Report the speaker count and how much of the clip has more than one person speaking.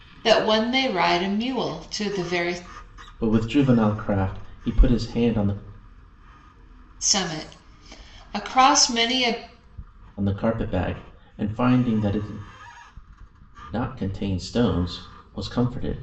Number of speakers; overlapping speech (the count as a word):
two, no overlap